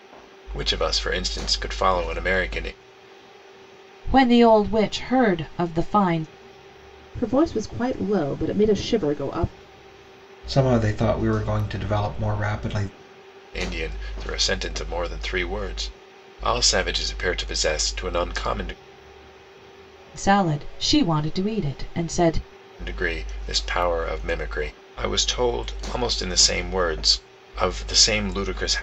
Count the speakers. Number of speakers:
four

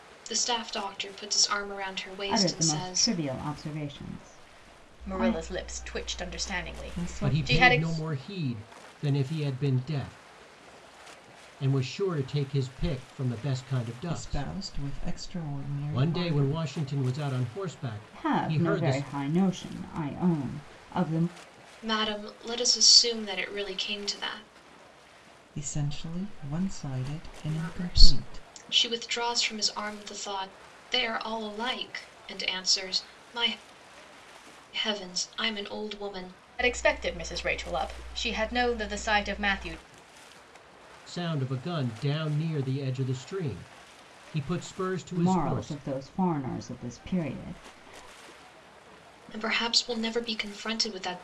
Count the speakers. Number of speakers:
five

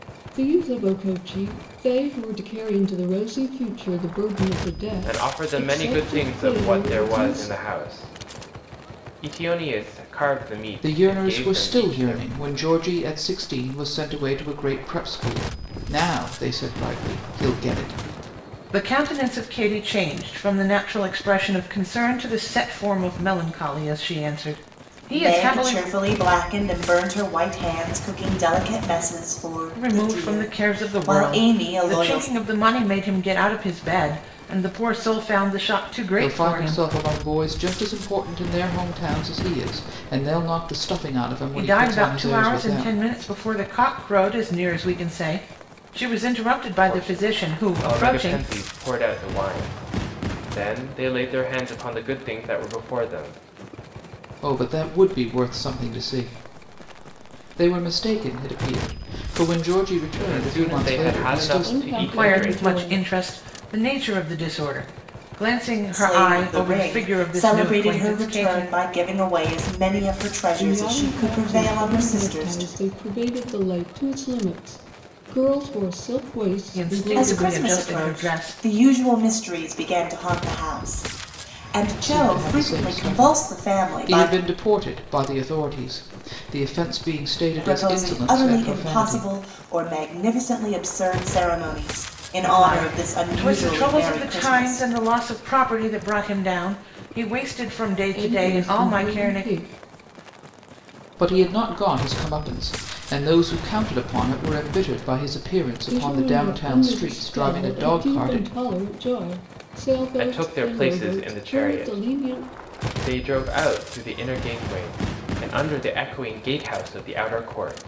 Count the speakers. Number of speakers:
five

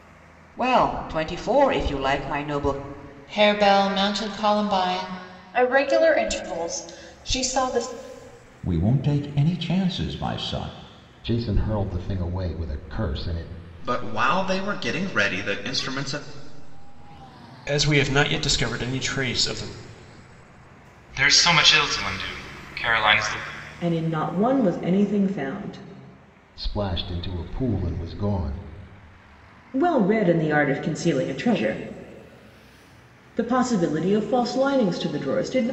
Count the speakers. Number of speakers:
nine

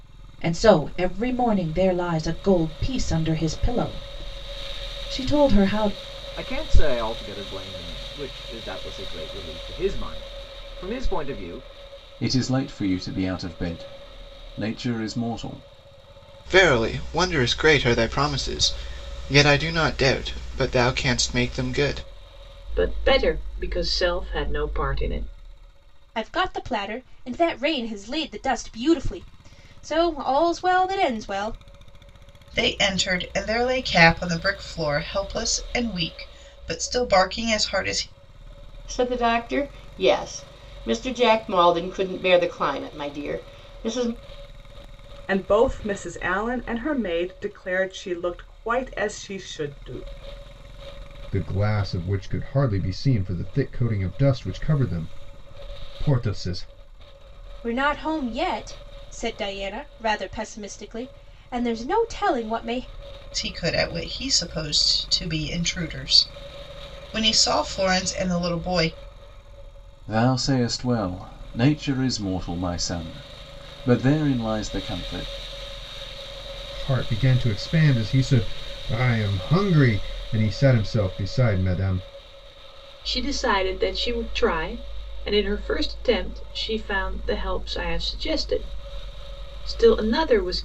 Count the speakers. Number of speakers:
ten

